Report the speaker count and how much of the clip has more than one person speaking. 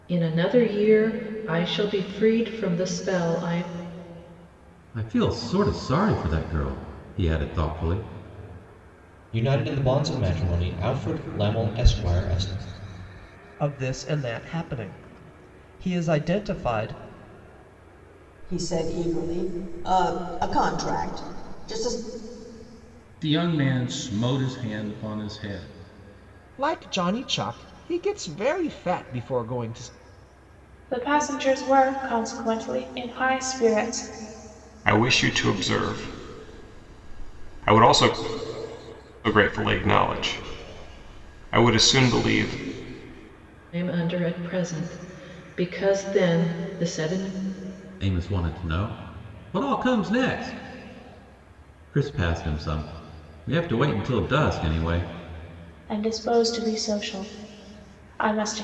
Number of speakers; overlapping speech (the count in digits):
9, no overlap